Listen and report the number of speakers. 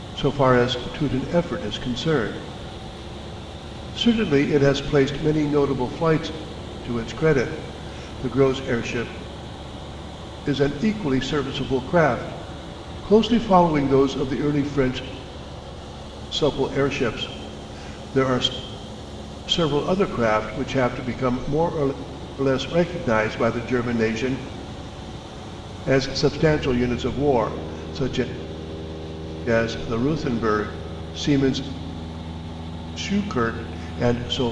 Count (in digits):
1